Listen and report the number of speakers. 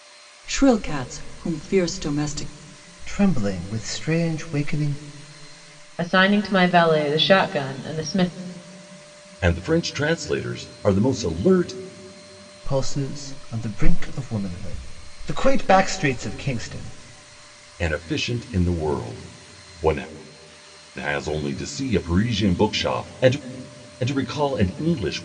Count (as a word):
four